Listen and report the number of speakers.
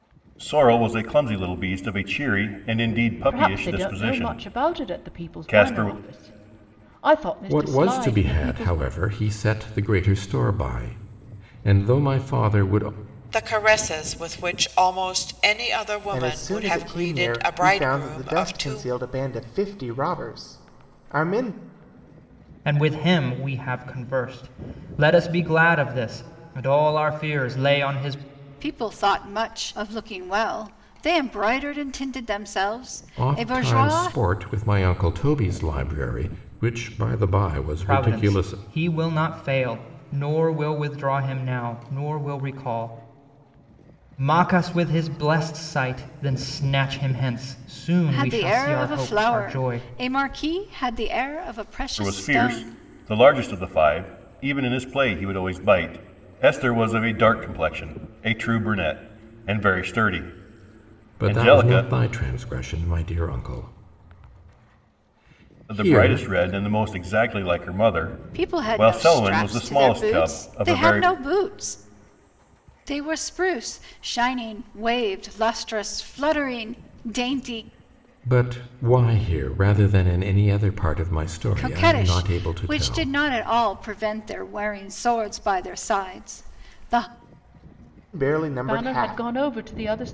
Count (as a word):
seven